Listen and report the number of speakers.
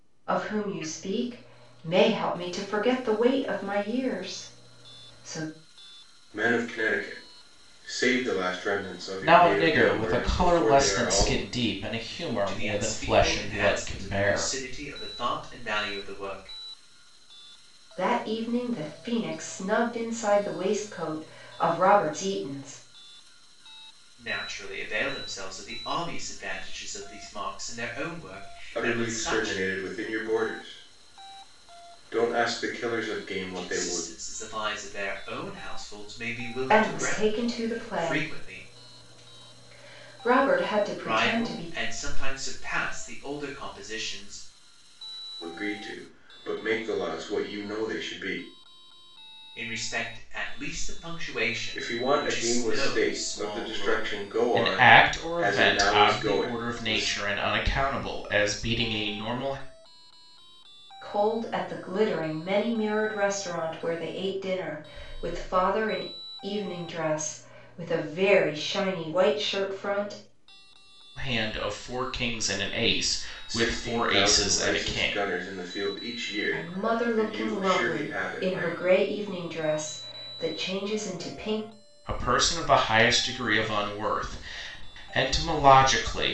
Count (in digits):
4